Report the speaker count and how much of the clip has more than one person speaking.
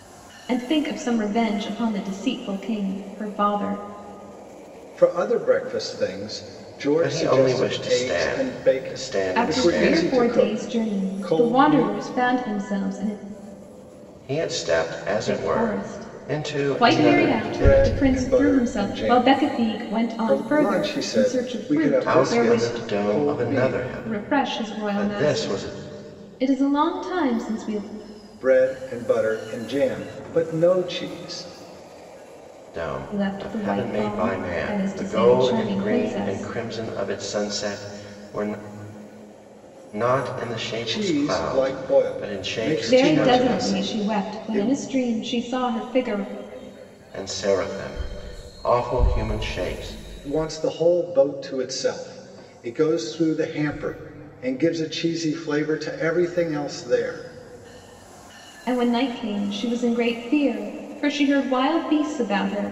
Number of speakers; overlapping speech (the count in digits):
3, about 36%